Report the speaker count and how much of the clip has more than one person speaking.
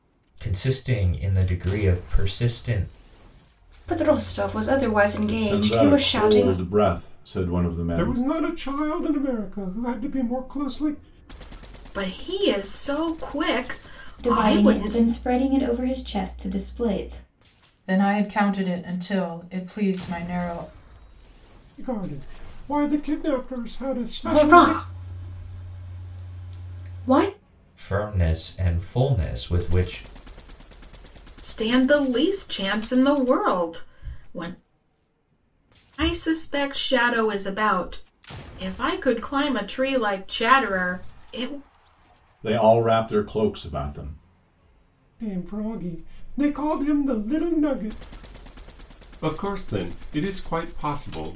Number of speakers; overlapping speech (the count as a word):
seven, about 6%